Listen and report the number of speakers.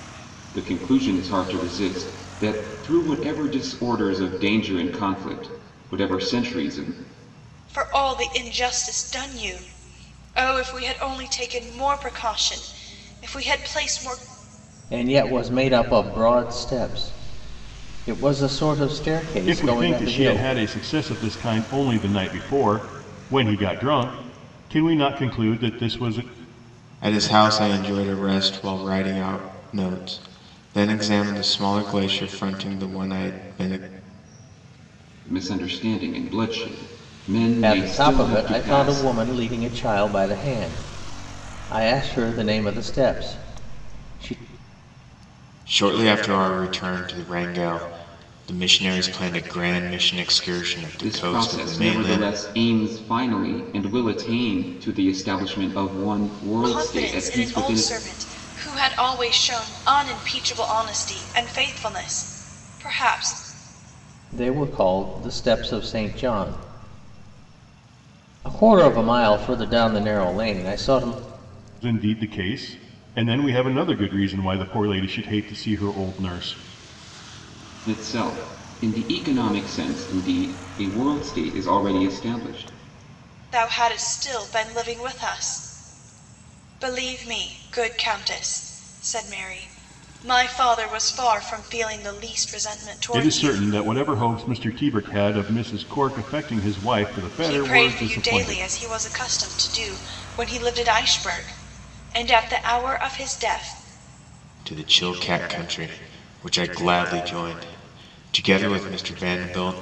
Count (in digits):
5